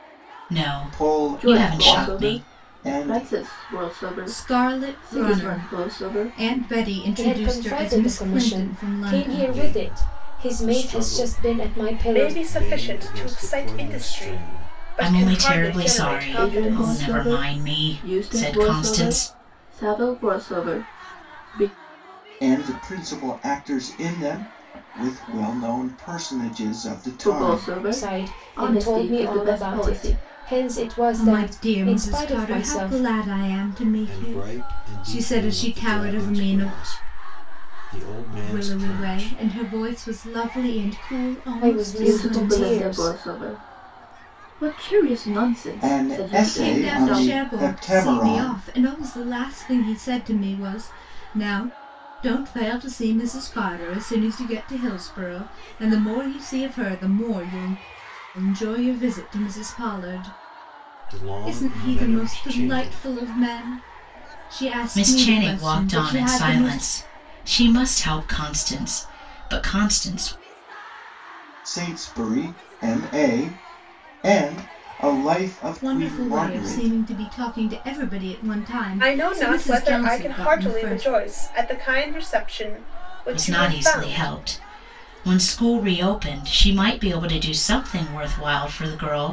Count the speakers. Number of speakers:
7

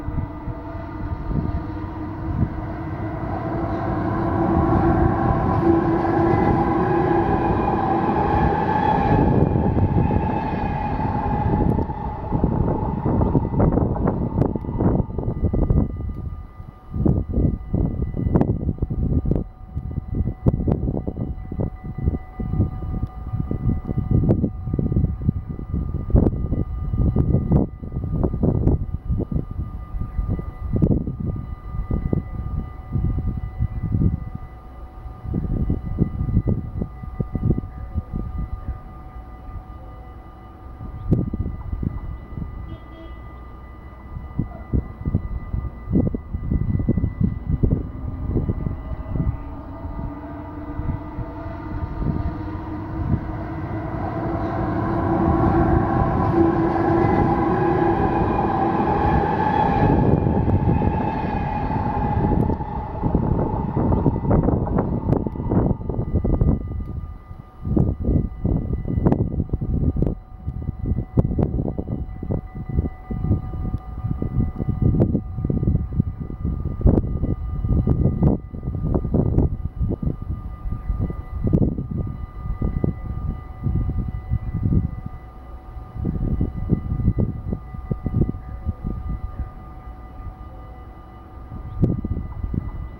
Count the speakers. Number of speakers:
0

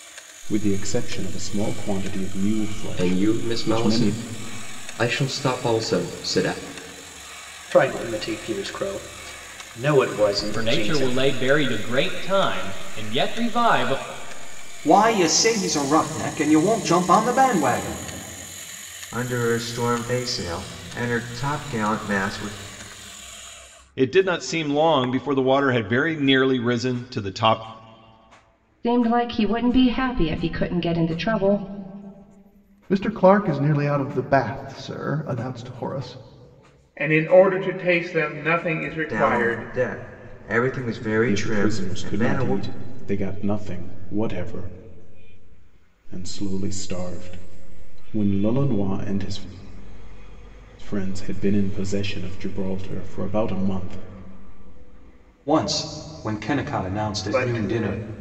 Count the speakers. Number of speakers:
10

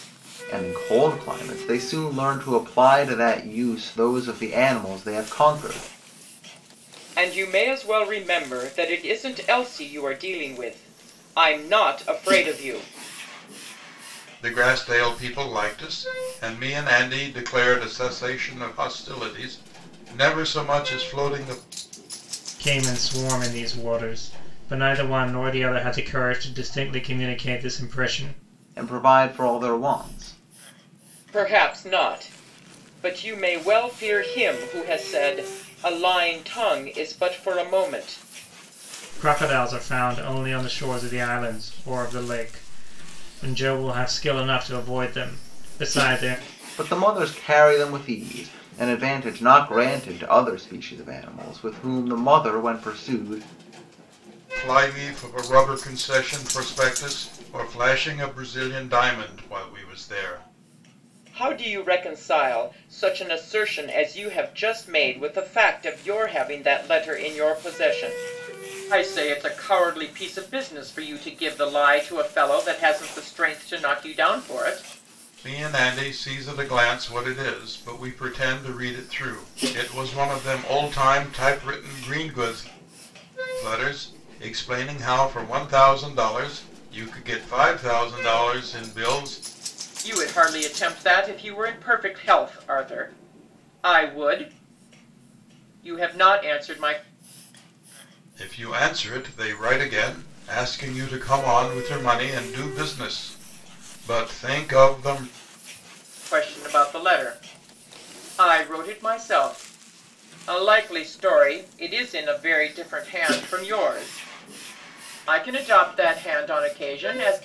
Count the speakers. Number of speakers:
4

